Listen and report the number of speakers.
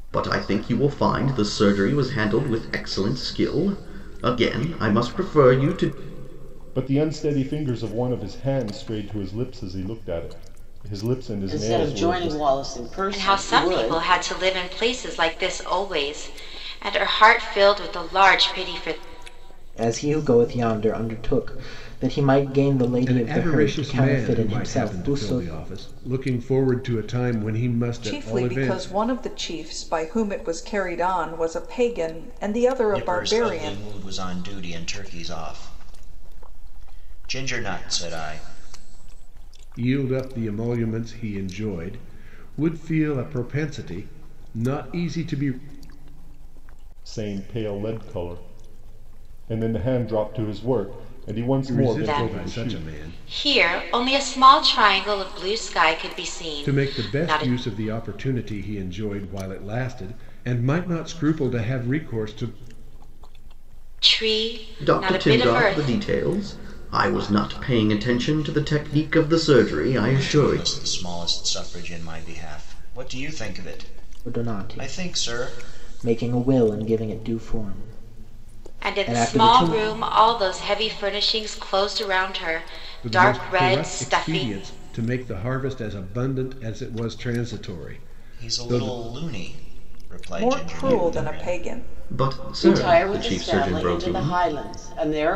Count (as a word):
eight